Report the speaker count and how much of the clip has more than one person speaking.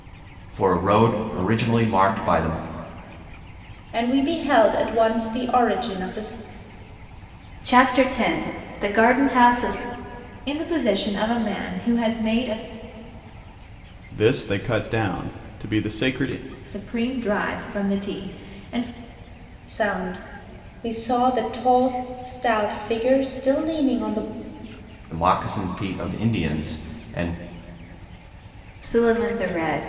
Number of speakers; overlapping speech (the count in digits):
5, no overlap